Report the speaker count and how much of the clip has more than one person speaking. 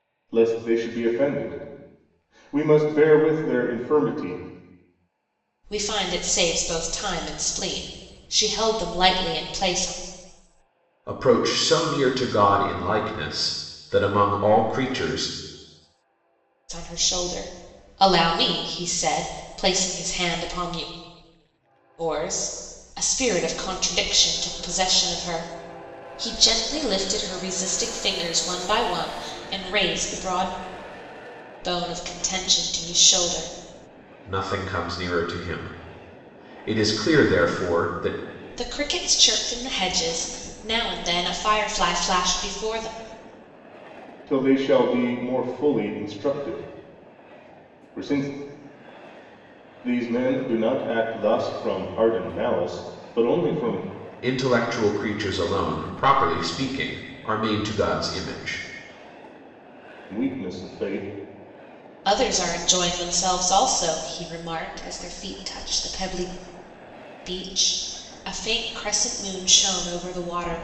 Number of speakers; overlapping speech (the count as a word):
three, no overlap